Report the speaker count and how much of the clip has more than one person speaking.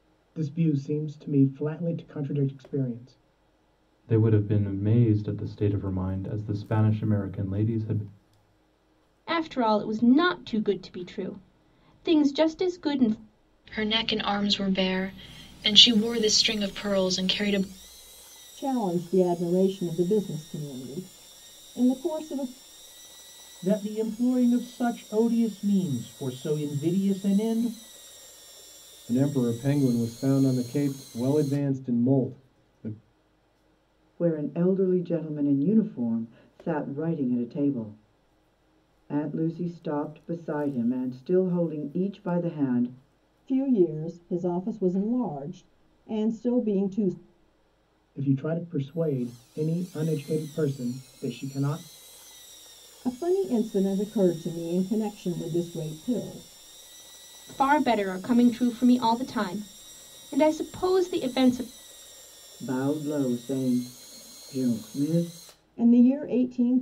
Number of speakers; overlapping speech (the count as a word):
eight, no overlap